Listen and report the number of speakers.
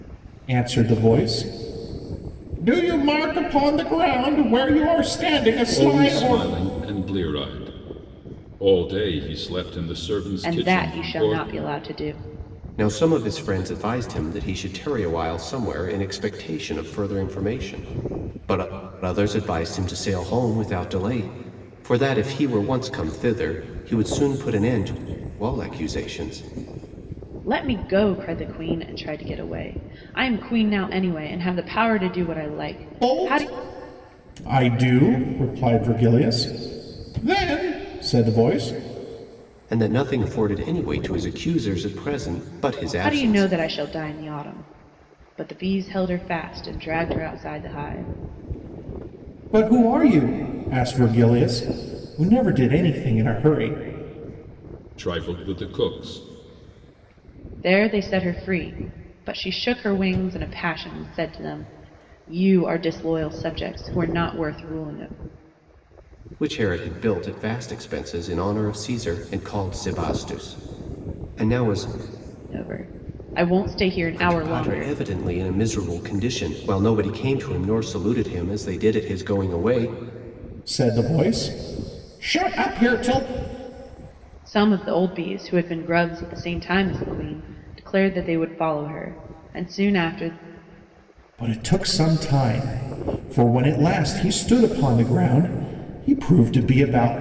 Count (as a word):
four